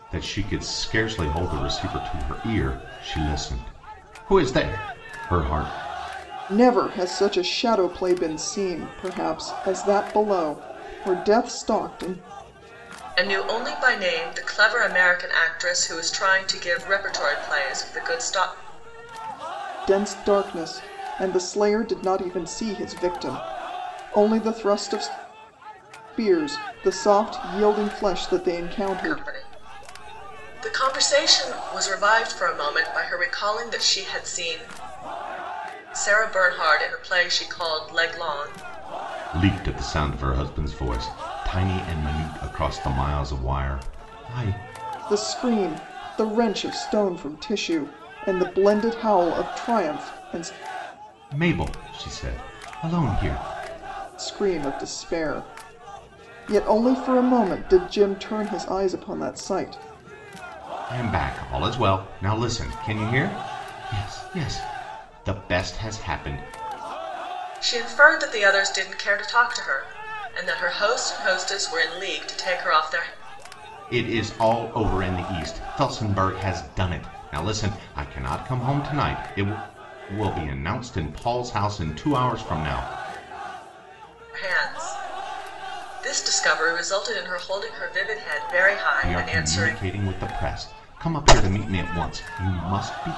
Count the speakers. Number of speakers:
three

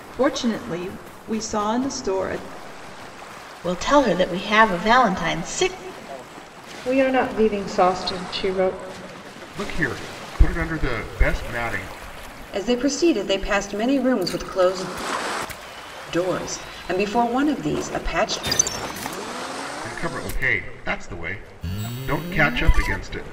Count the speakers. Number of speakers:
five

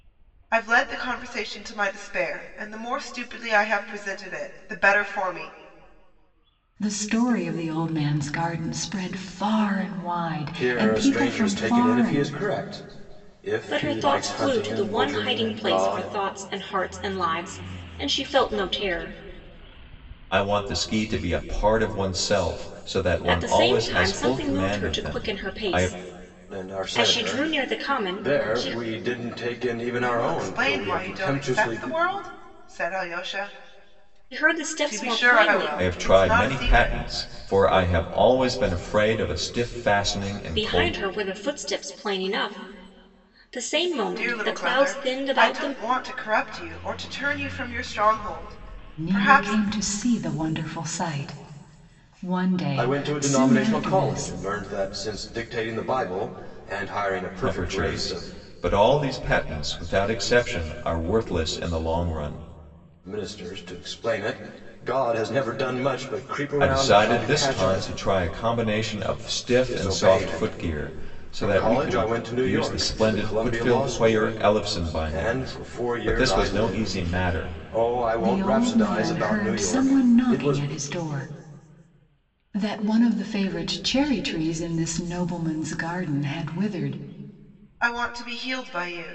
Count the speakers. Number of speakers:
five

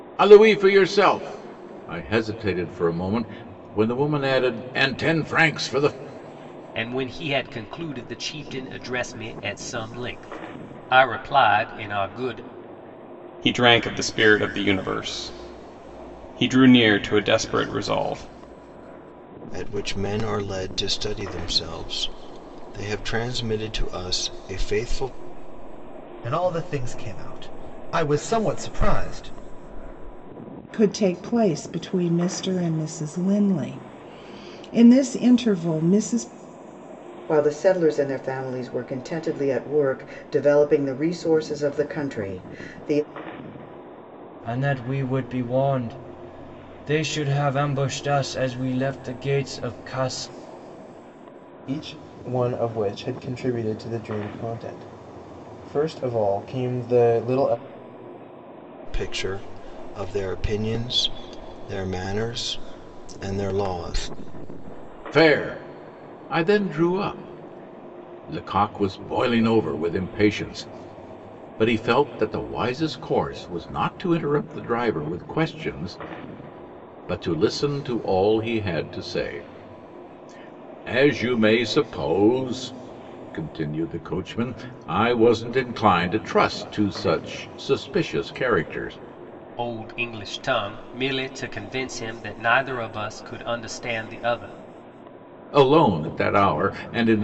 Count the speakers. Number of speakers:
nine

